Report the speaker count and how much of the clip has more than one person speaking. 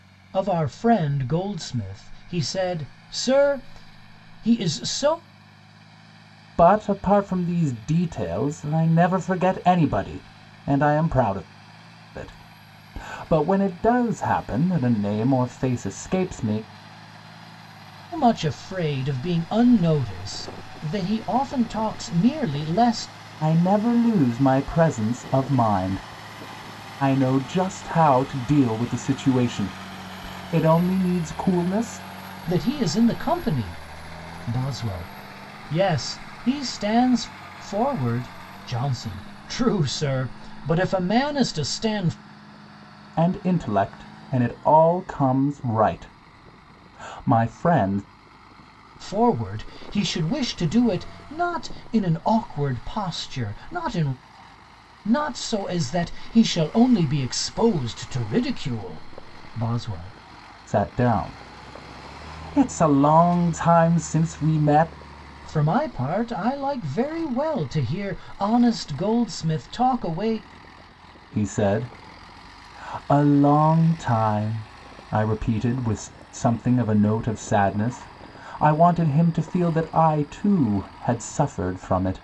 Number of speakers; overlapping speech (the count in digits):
2, no overlap